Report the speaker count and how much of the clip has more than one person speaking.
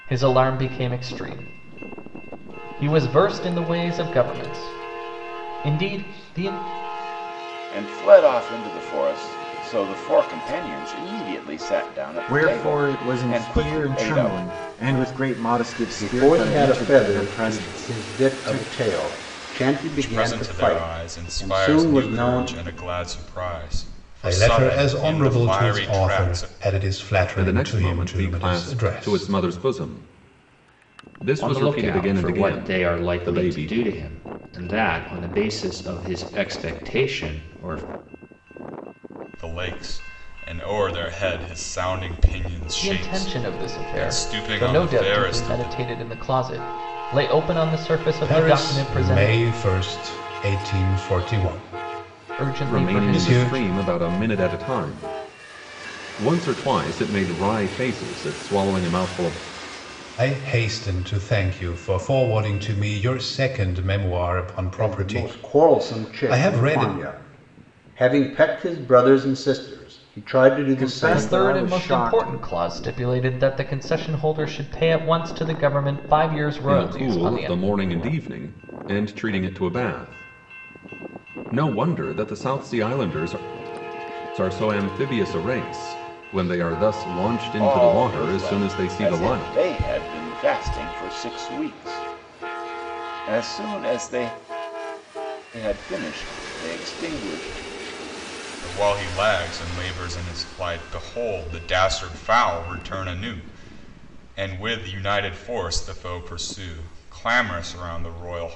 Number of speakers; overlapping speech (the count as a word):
eight, about 25%